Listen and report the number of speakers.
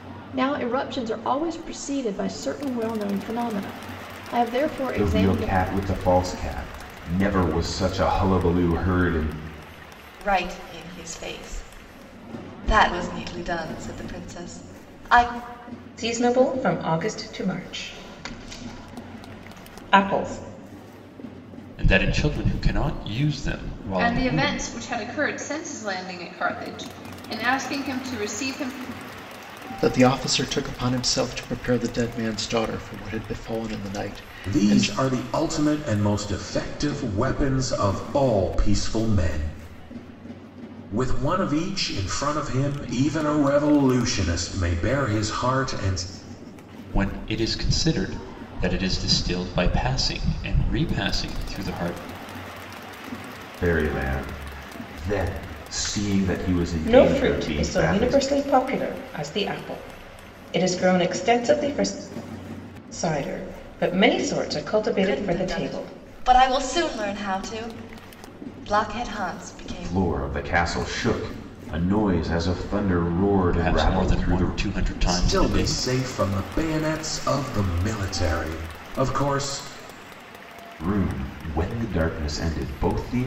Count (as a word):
eight